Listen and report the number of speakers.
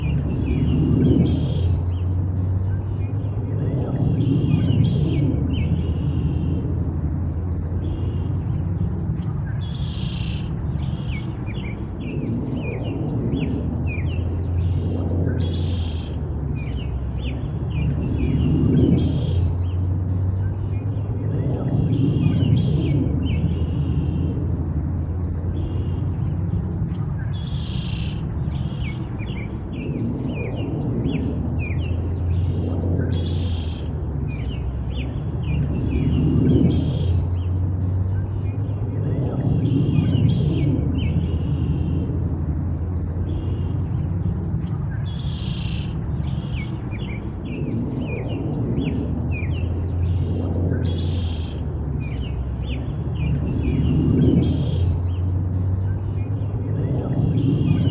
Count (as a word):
zero